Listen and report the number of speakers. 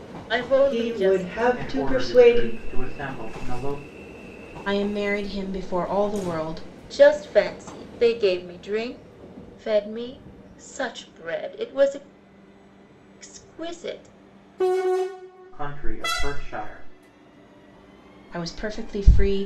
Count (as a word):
four